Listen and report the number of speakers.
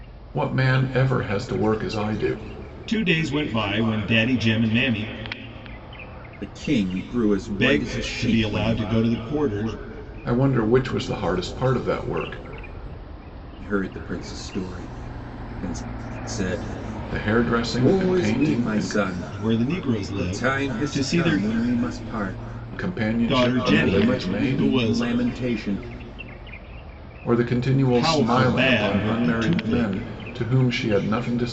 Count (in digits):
3